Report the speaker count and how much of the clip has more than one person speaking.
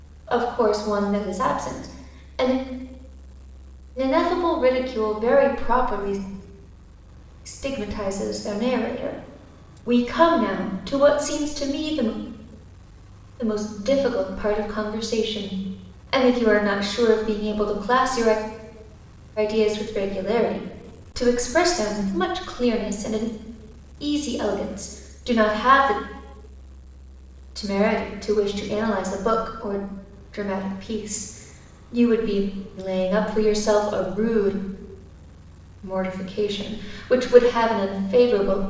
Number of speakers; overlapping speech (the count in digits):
1, no overlap